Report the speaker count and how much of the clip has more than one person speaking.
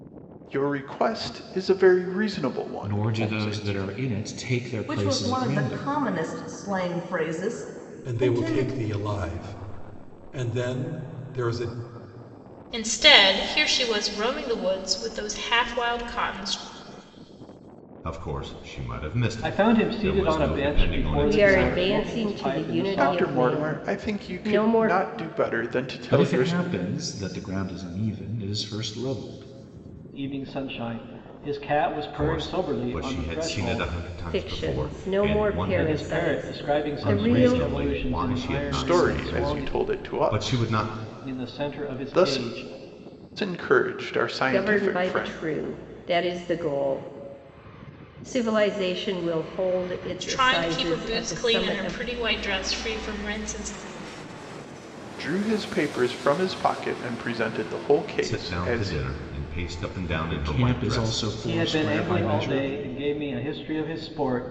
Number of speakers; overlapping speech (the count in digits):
8, about 39%